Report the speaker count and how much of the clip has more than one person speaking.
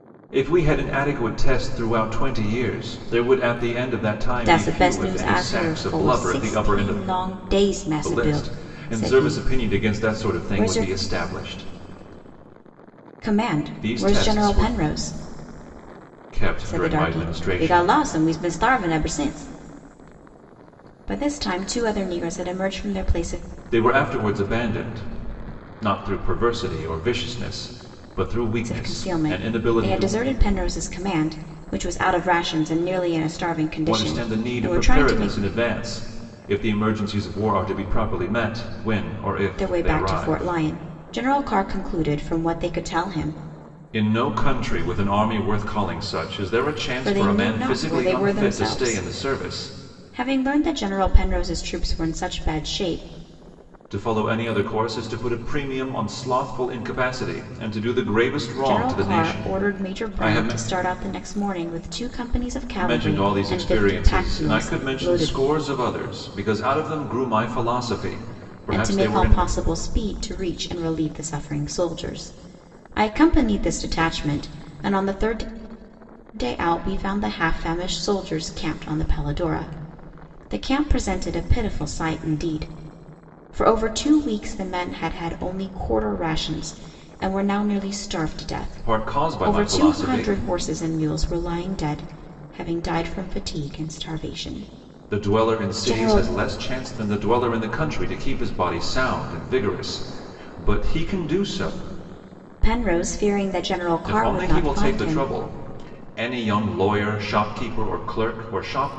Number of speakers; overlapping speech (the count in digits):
2, about 23%